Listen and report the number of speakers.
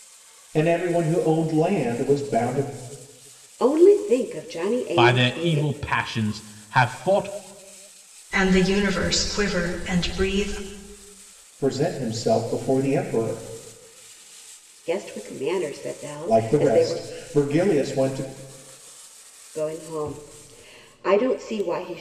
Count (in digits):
4